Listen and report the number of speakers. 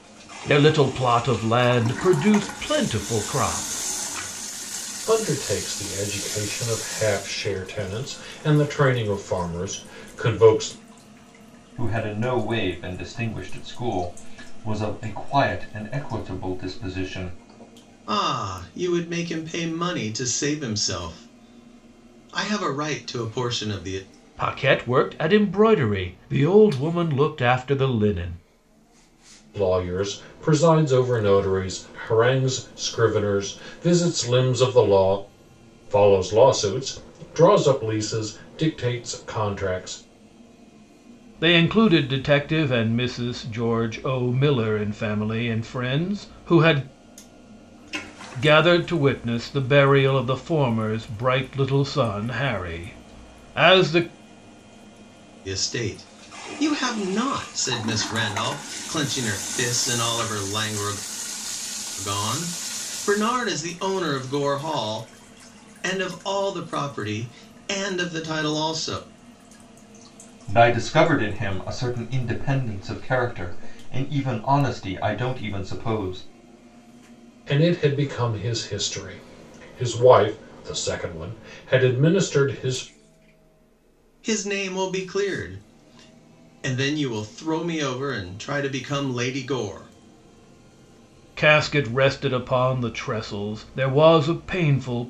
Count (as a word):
four